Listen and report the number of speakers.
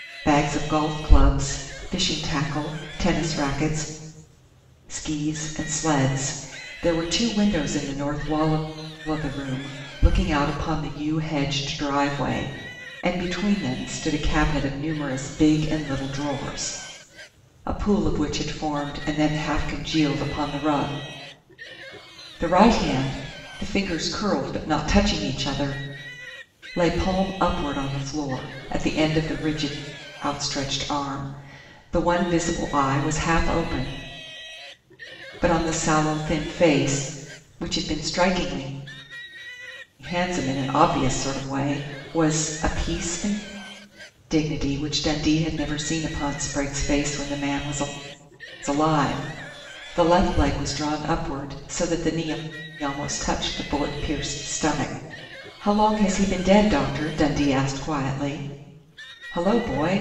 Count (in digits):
1